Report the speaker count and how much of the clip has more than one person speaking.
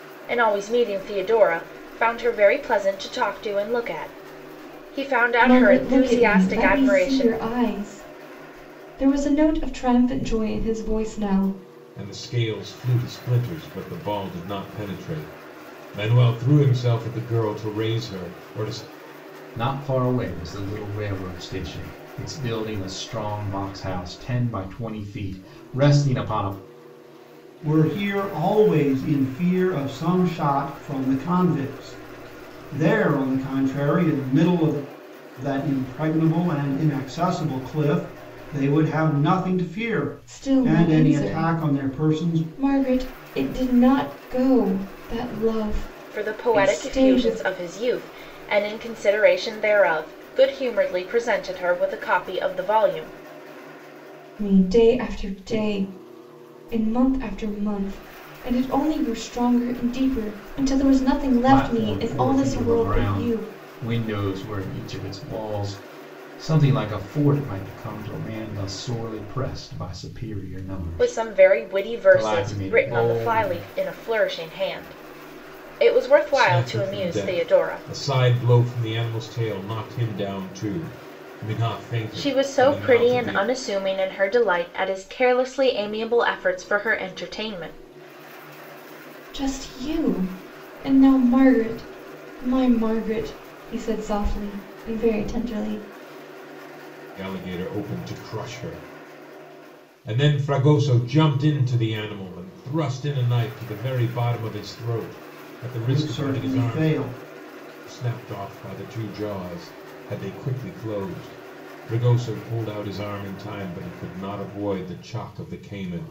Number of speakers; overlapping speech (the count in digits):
5, about 12%